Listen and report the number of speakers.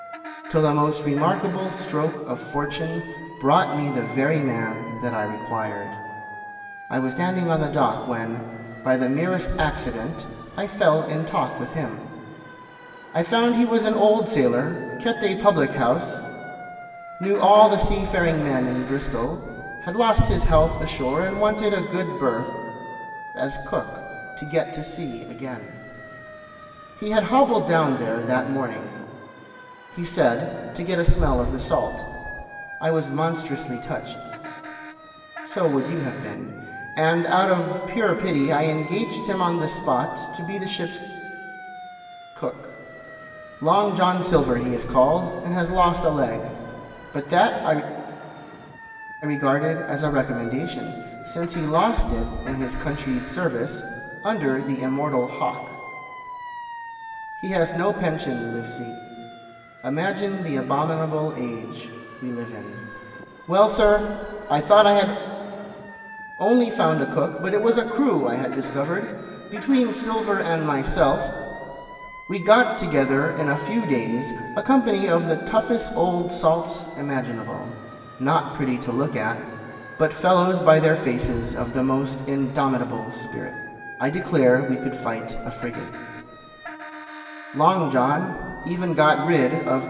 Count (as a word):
one